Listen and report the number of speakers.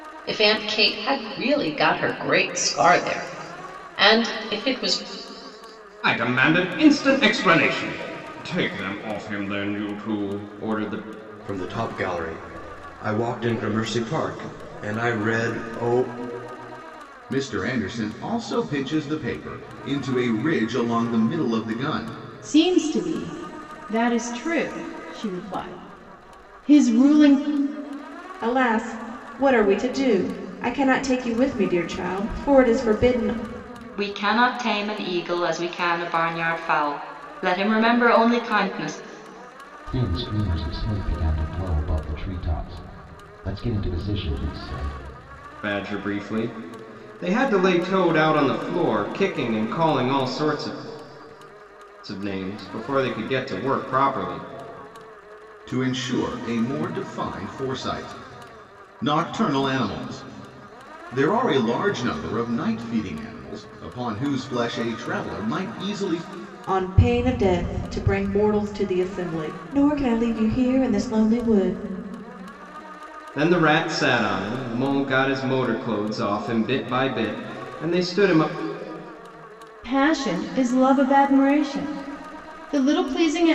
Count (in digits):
8